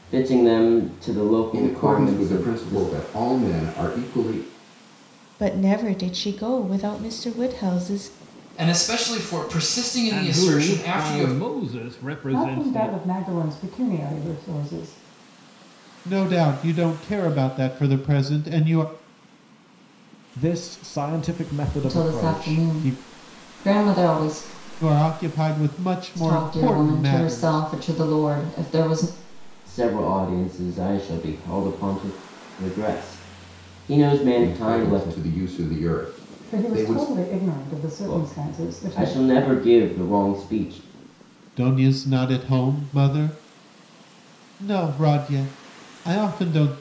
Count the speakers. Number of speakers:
nine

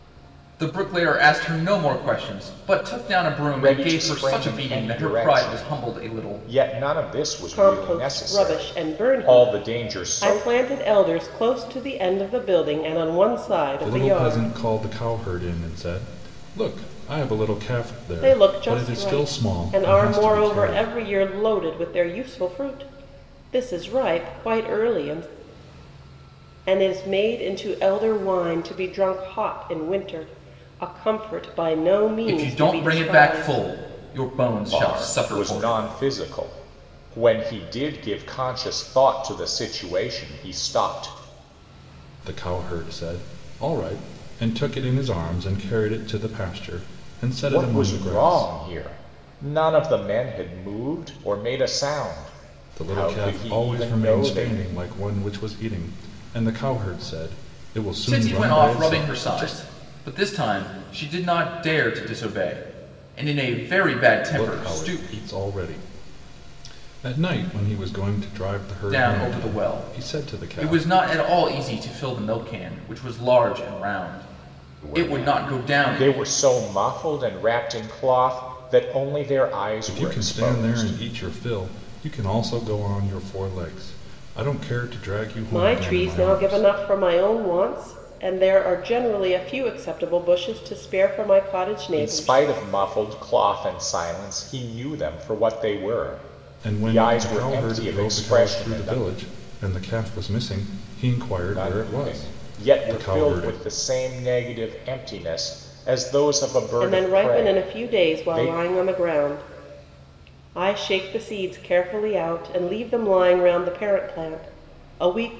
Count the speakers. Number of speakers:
four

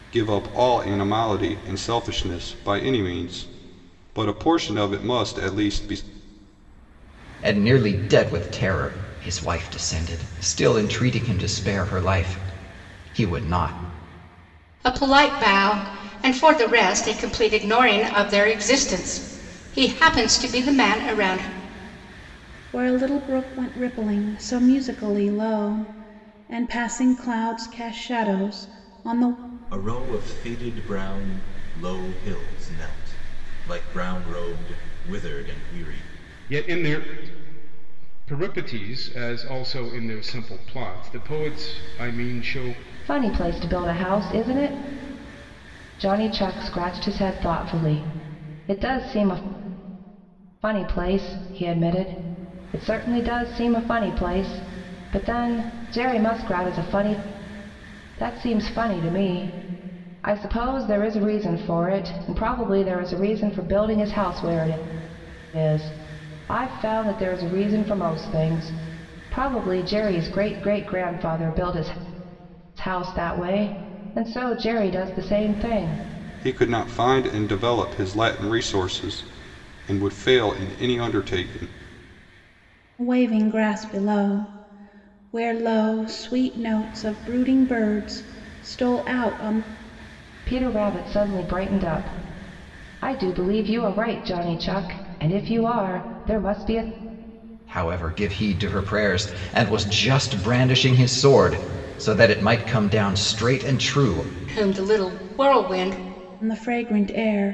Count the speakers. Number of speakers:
seven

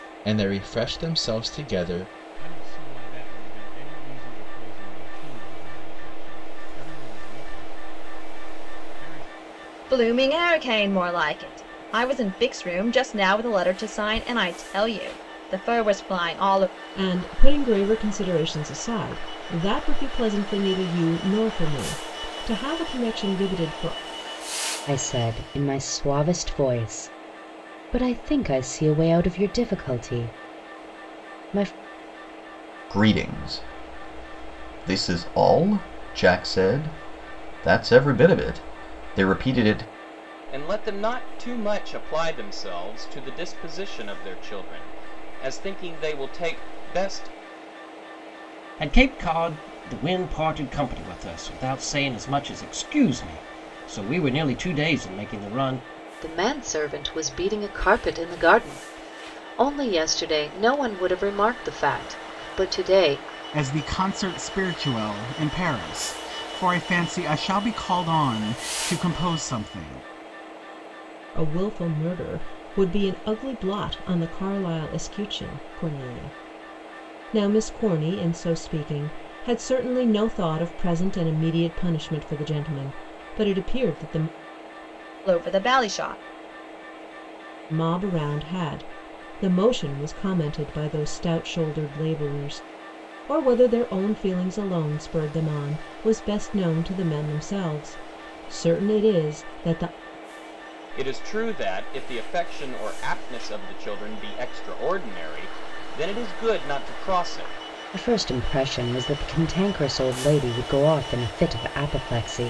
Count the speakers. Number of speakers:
ten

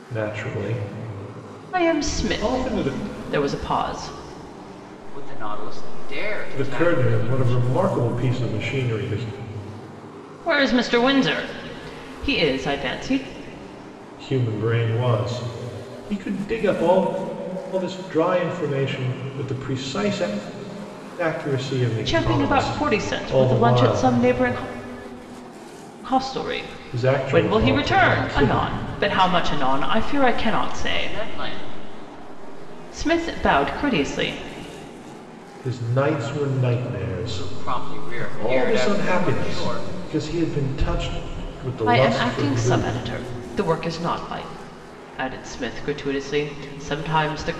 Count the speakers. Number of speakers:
three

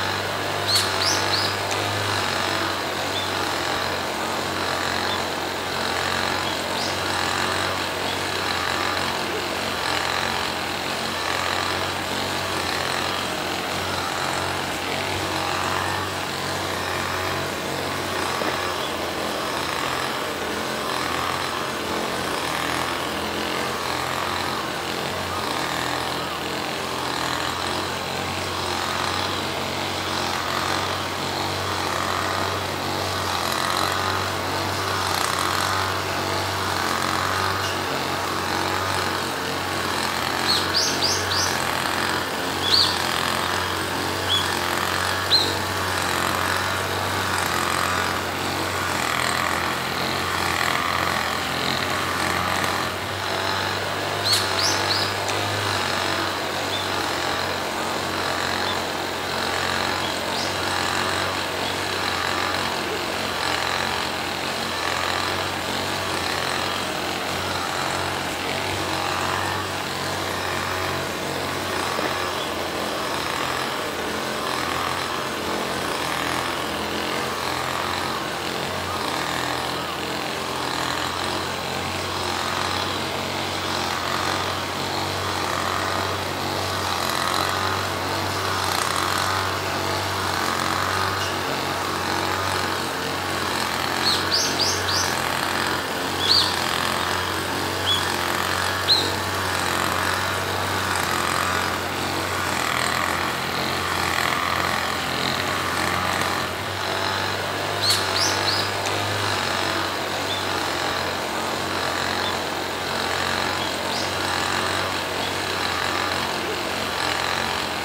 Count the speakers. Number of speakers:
zero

